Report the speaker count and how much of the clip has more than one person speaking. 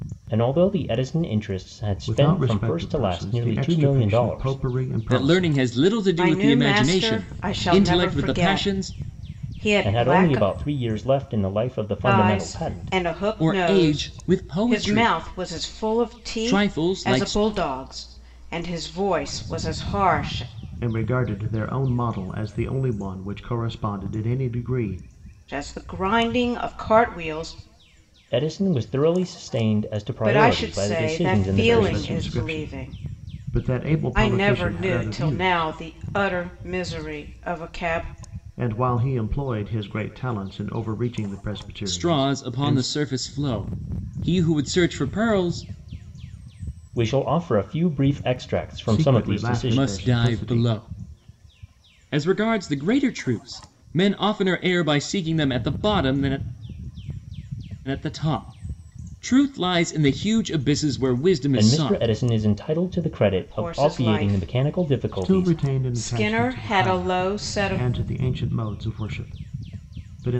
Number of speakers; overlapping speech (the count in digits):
4, about 34%